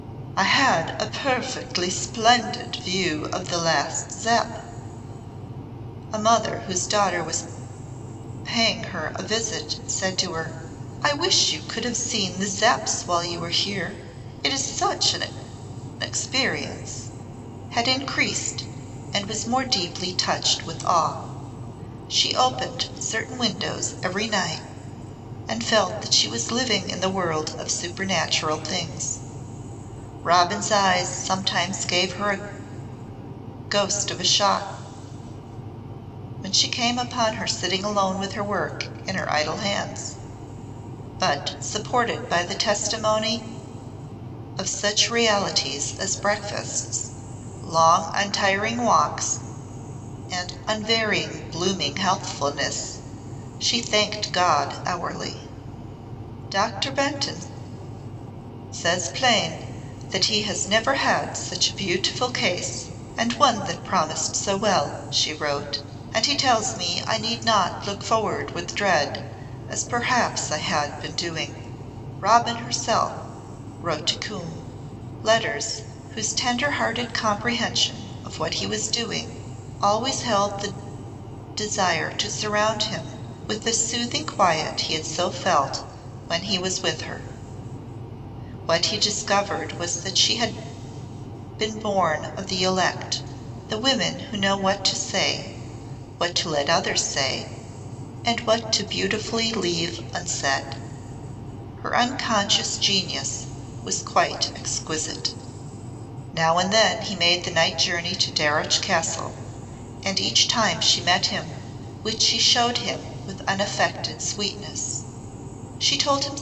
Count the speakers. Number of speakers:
1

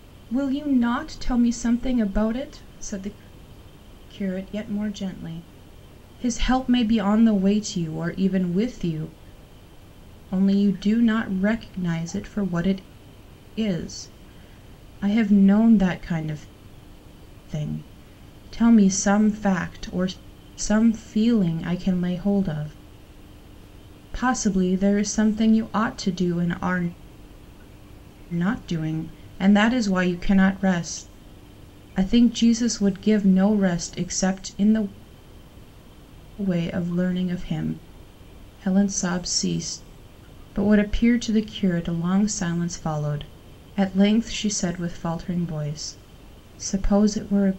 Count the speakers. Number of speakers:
1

